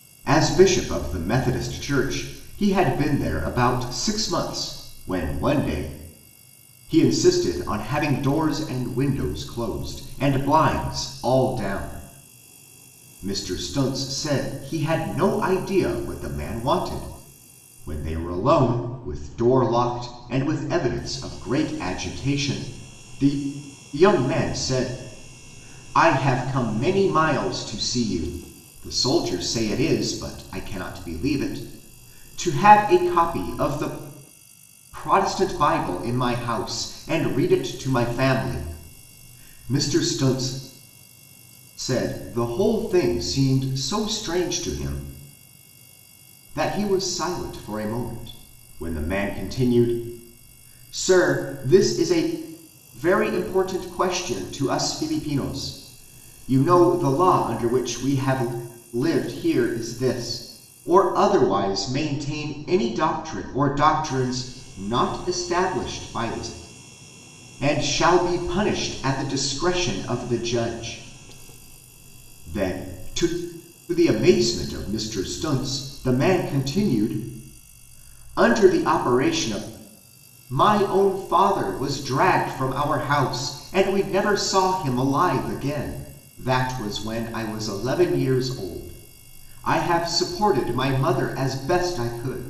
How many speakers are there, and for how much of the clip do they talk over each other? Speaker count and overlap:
1, no overlap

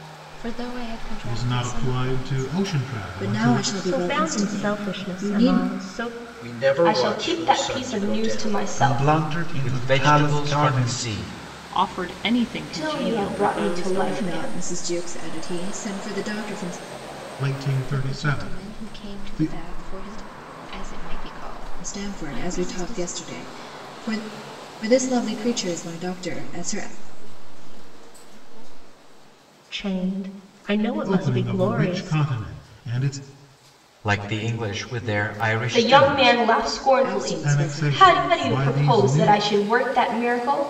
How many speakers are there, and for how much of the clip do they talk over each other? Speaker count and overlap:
10, about 46%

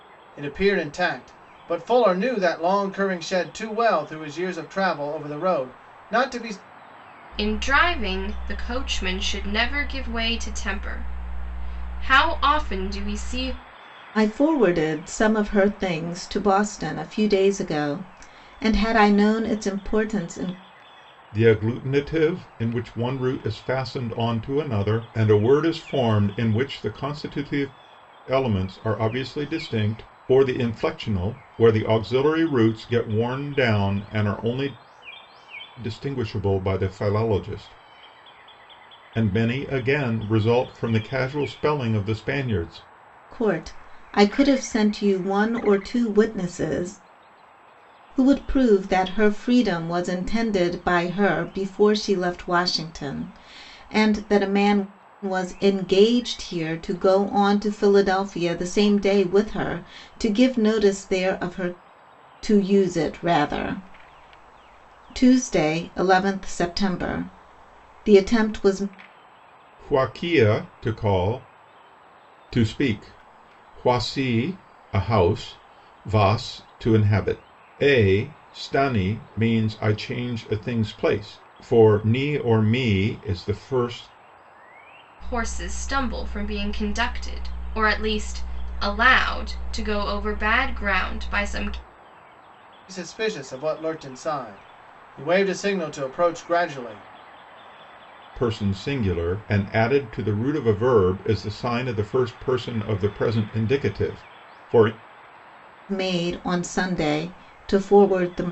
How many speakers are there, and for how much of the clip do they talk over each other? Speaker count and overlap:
4, no overlap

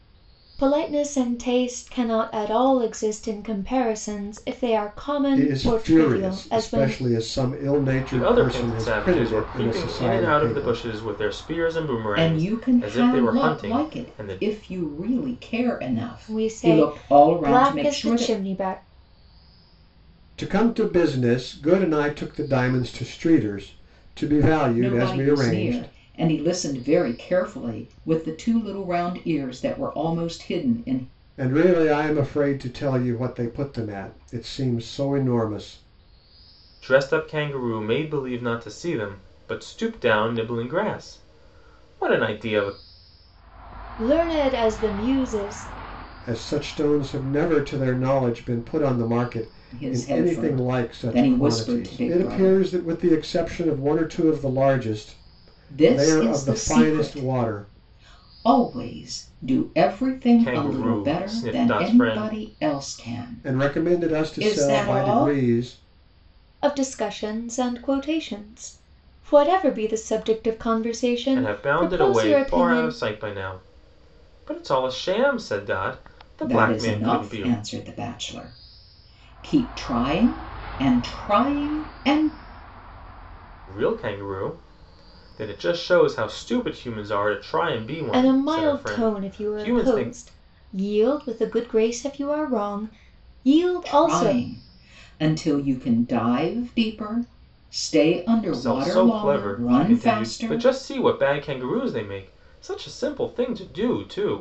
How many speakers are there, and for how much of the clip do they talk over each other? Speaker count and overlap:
4, about 25%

